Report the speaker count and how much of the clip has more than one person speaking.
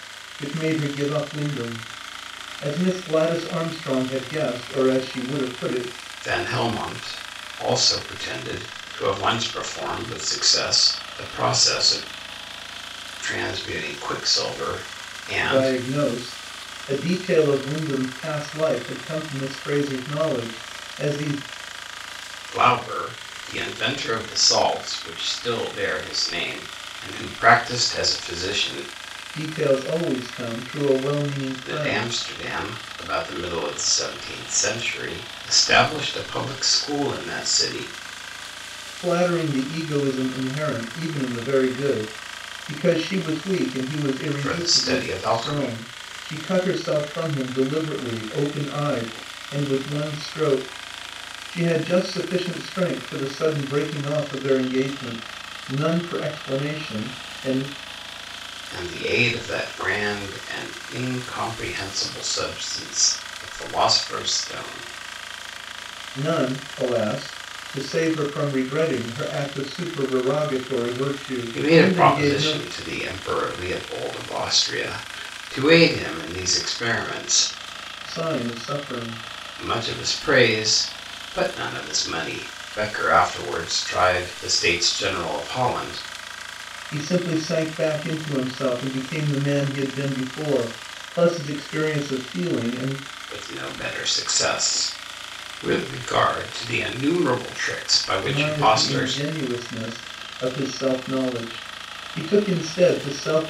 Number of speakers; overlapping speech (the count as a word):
two, about 4%